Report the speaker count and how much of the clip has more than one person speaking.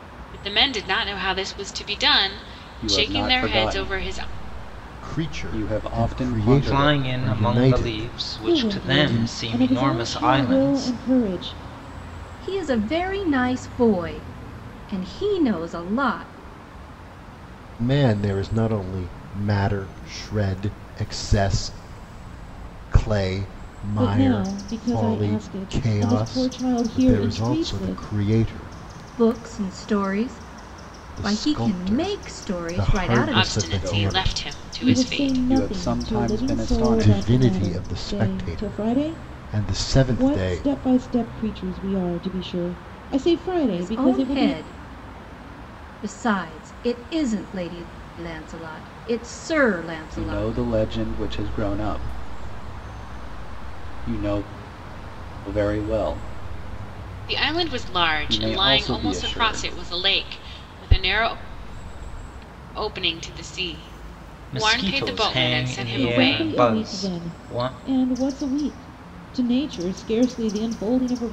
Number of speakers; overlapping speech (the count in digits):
6, about 38%